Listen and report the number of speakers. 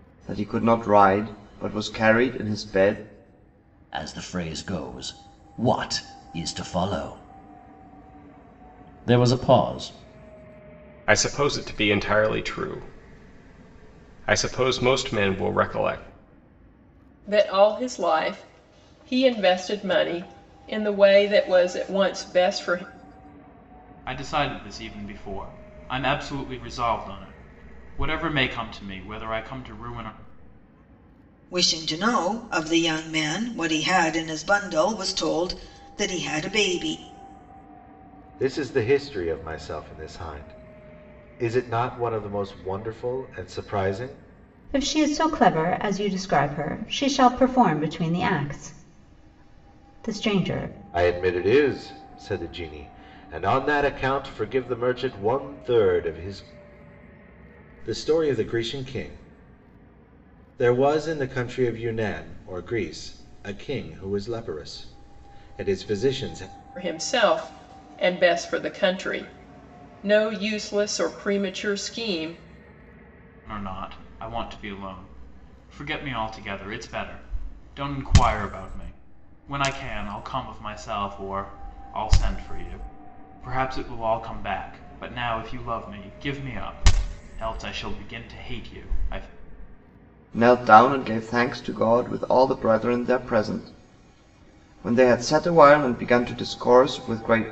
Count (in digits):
8